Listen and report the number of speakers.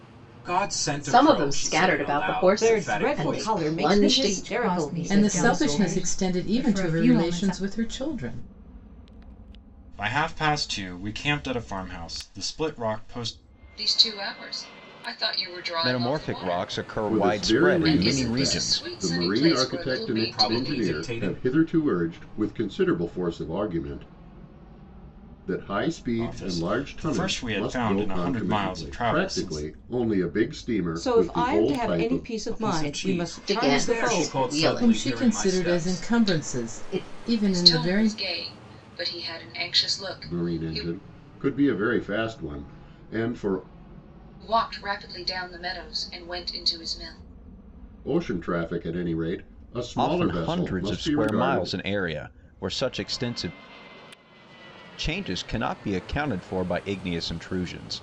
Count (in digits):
9